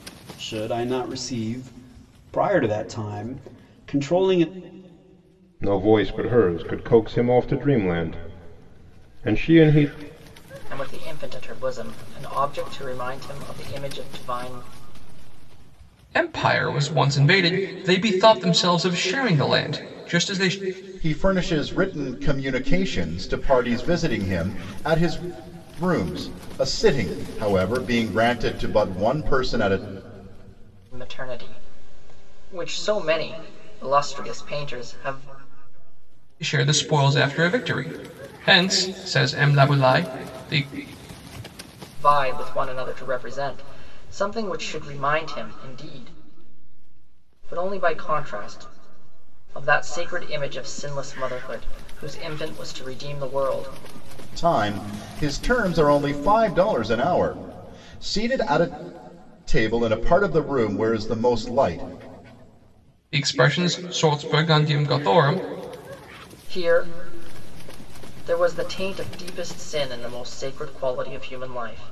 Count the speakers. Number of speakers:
five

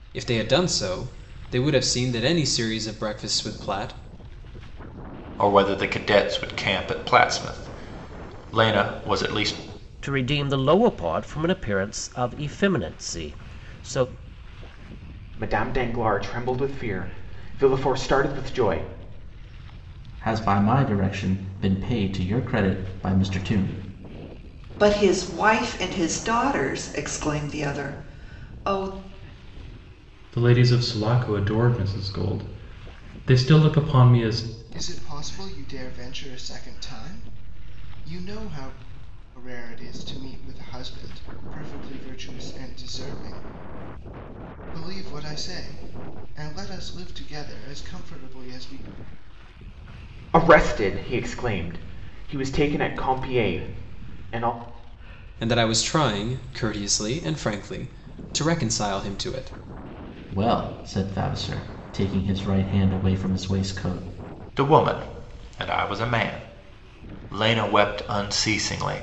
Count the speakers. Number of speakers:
eight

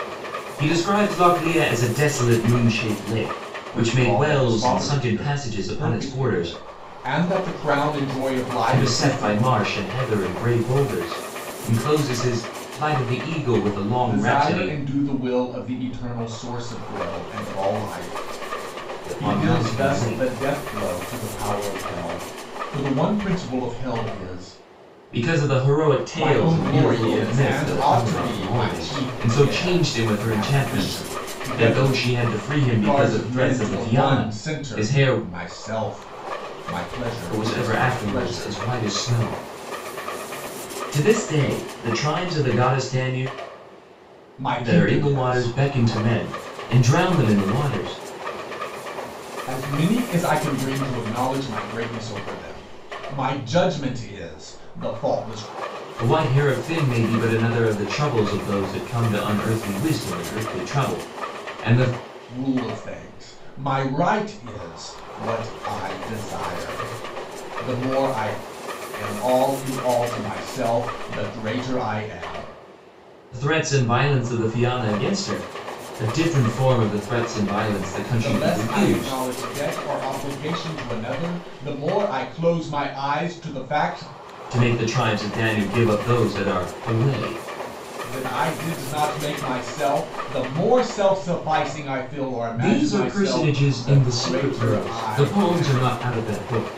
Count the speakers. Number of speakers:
two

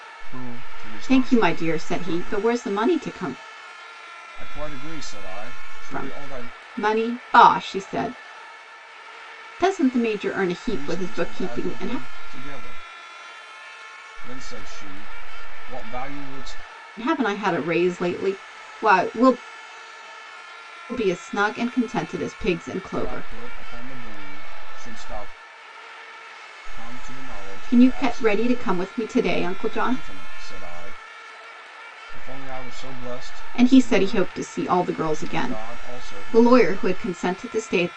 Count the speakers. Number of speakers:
two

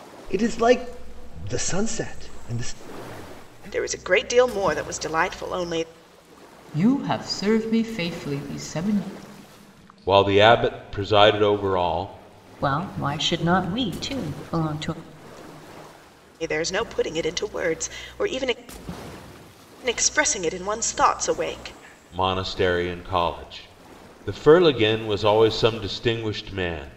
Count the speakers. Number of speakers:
five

